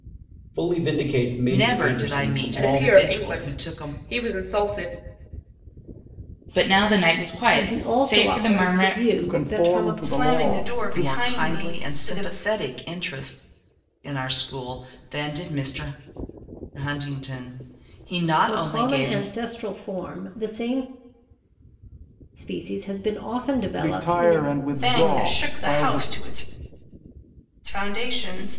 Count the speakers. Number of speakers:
7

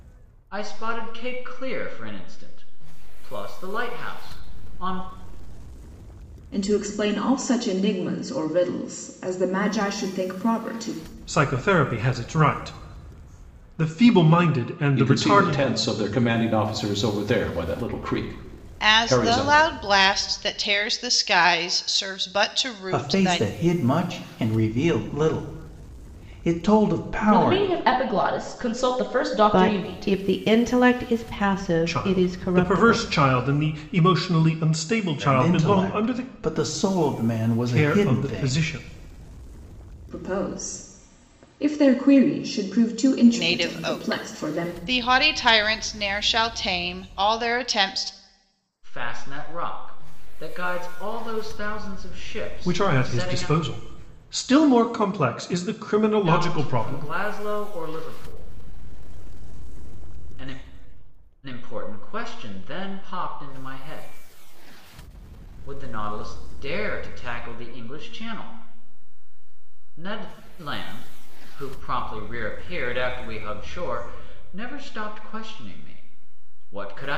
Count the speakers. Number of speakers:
8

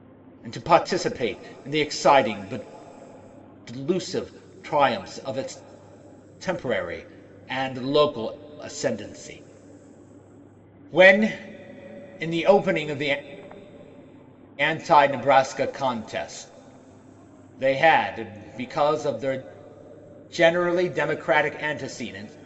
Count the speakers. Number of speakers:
1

